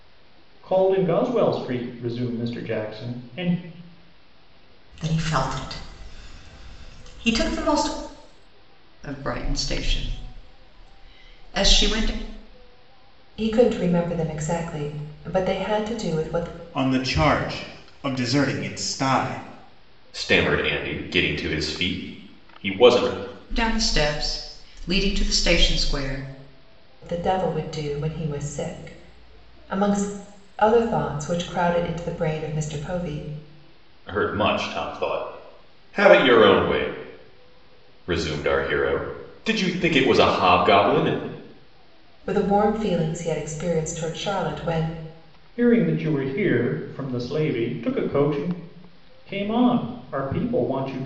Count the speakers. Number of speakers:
six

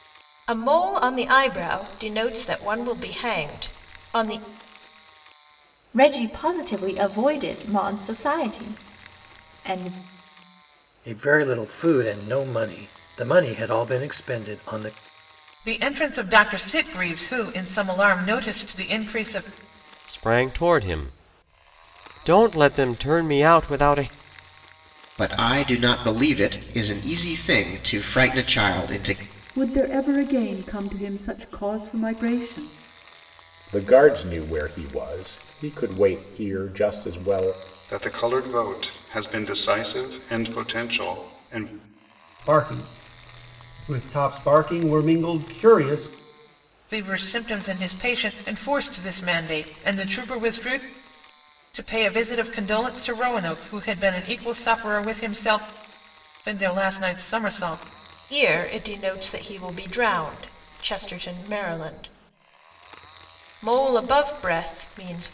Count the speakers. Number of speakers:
ten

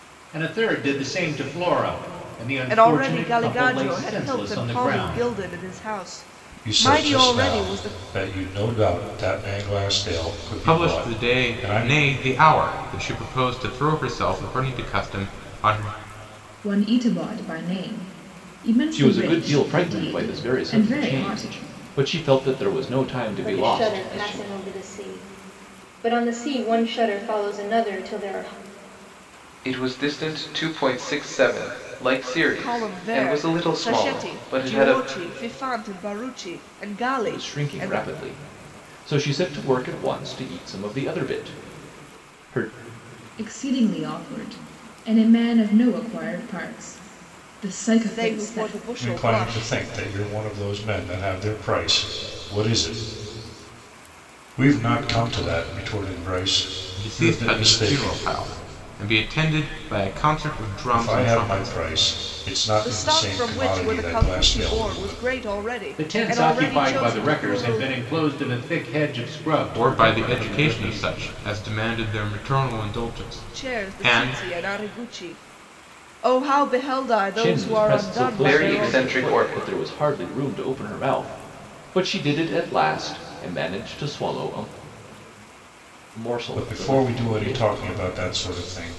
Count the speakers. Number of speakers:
eight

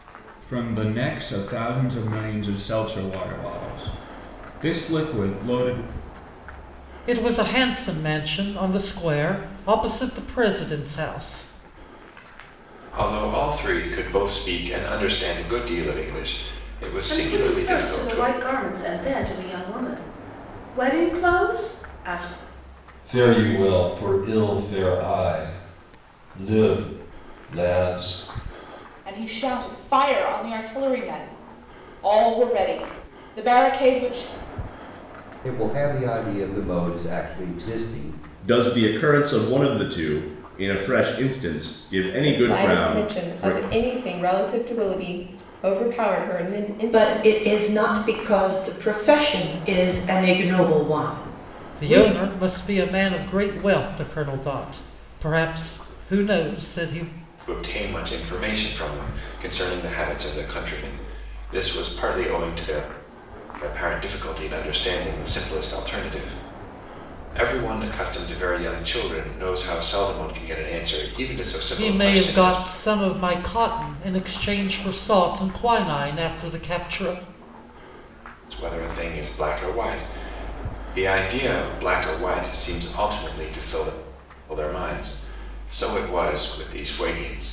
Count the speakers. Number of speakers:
ten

